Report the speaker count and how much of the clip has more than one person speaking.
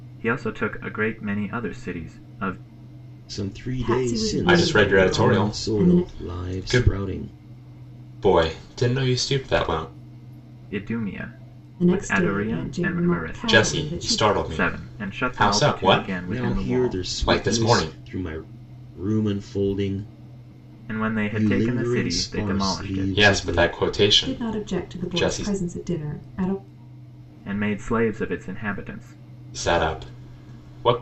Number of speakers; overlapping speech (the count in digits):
4, about 42%